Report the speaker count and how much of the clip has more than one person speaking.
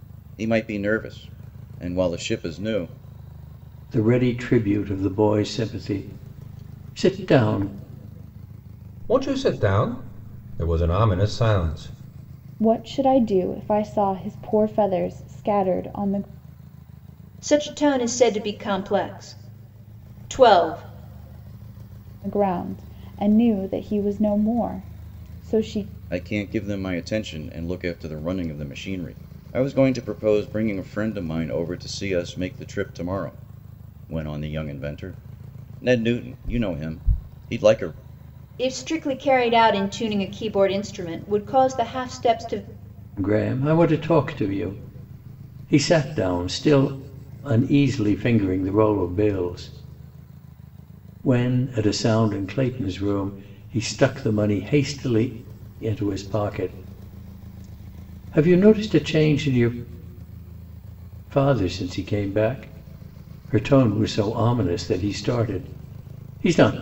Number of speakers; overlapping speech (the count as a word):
five, no overlap